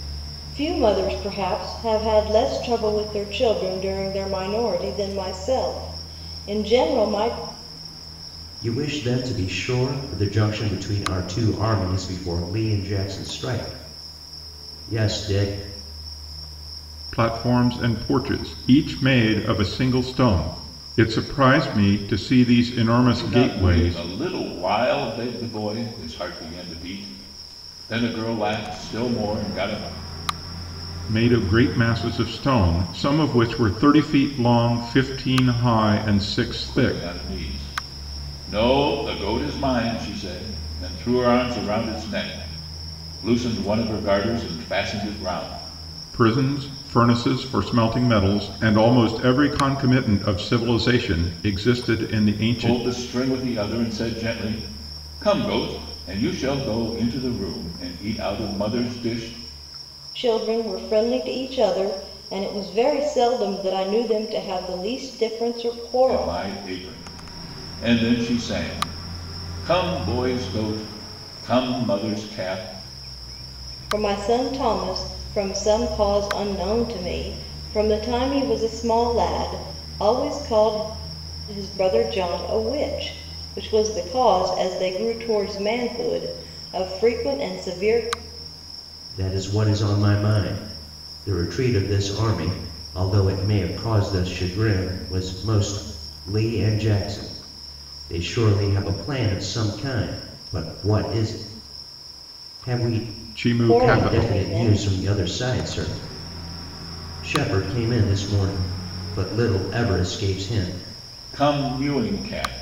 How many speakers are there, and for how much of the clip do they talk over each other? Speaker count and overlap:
four, about 3%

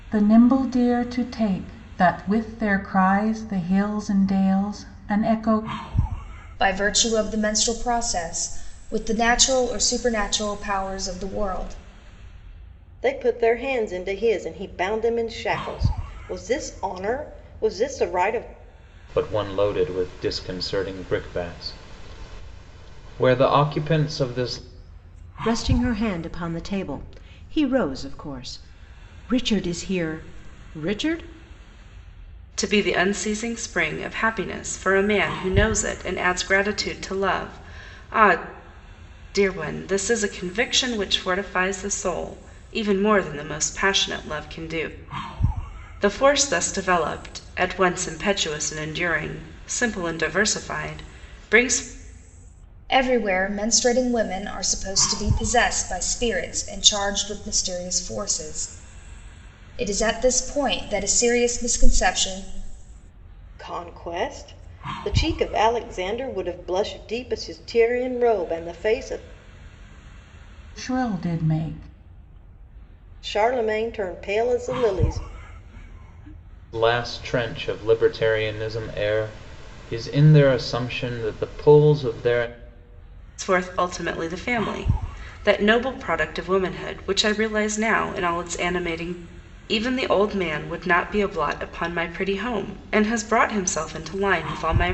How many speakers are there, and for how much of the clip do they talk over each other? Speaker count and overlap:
six, no overlap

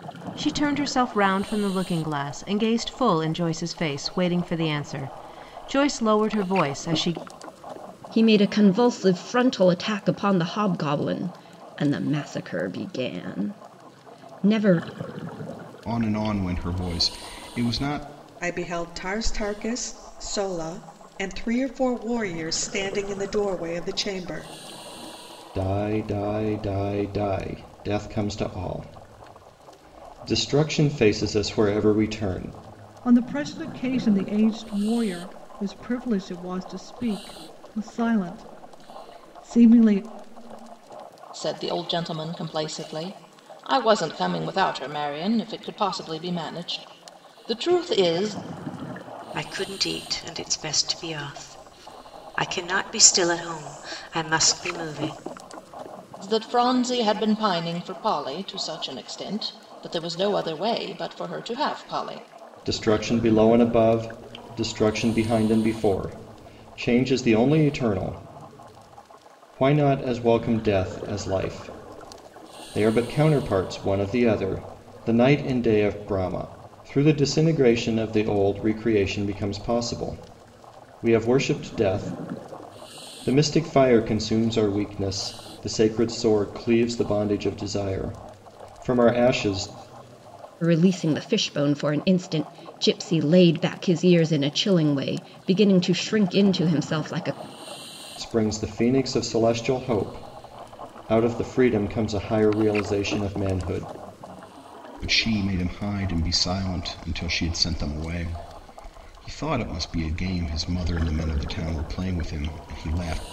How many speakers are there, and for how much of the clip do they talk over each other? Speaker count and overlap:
eight, no overlap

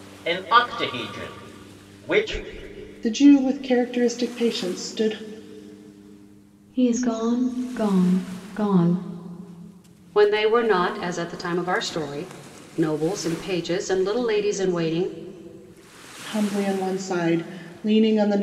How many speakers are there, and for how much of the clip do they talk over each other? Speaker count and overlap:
four, no overlap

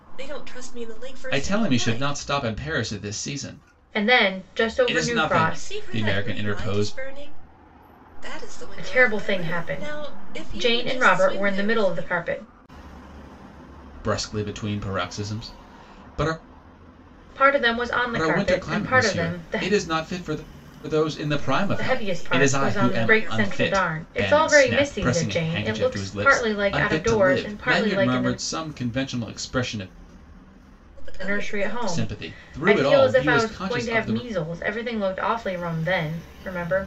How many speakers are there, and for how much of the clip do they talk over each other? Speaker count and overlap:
three, about 47%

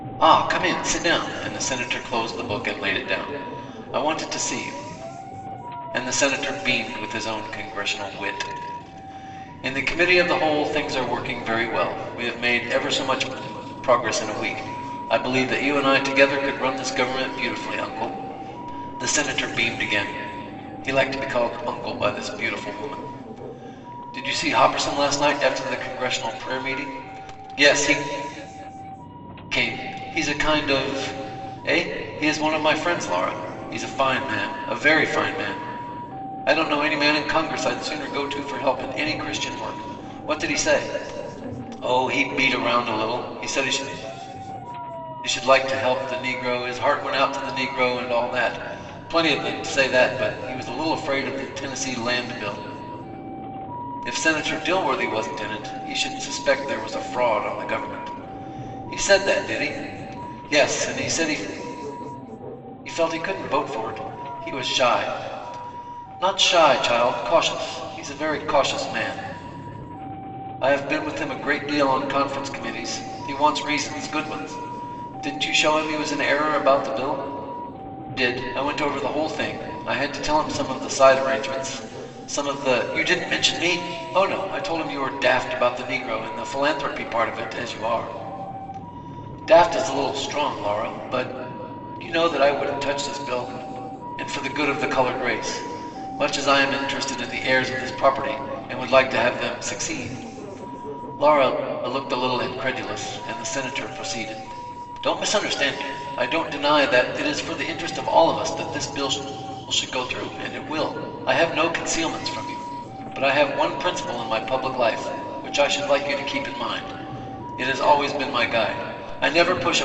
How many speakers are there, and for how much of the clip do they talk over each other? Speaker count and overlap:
one, no overlap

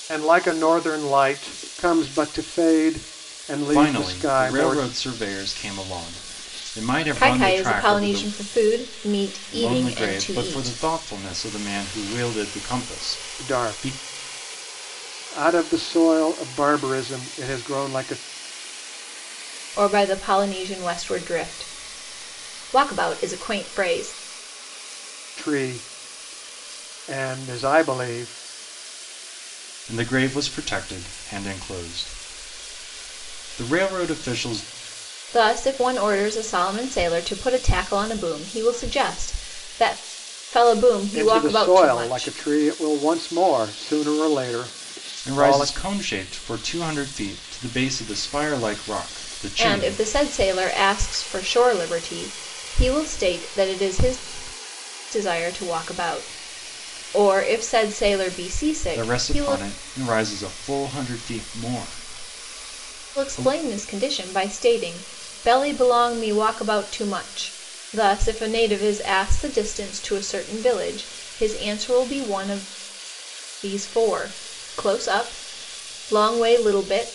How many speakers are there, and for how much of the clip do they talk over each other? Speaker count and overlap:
three, about 10%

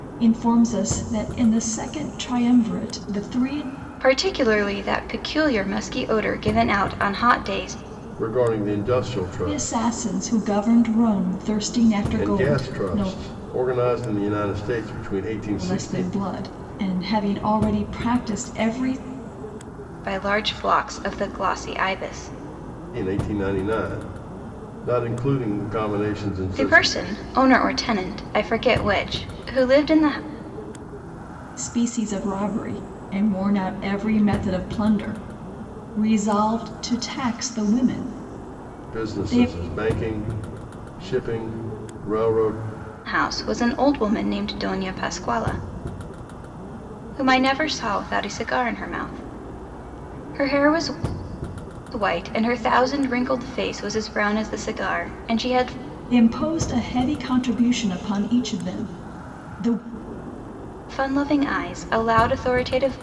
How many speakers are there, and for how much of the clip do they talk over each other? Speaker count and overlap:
three, about 5%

